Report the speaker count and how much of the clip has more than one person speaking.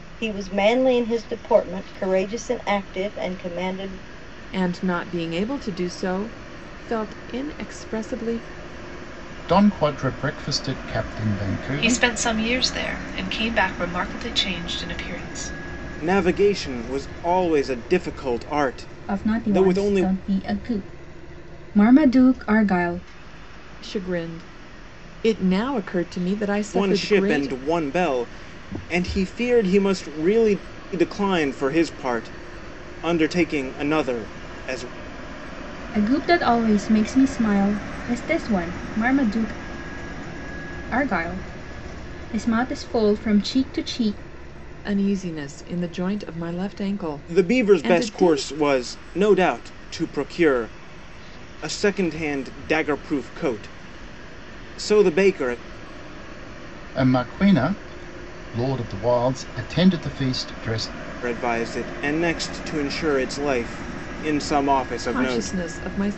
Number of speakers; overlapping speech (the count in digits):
6, about 6%